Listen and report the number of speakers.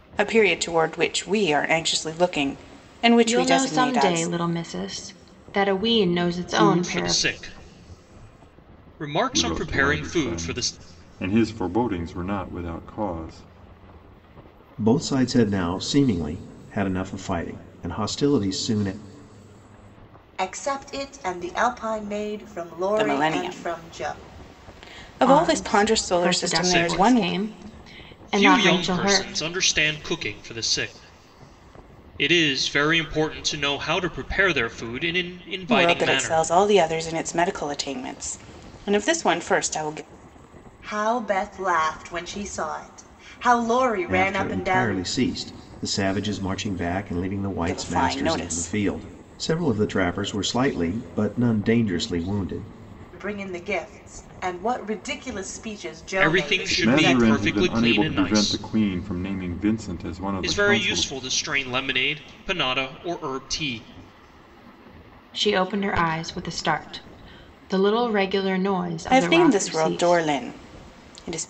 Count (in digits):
6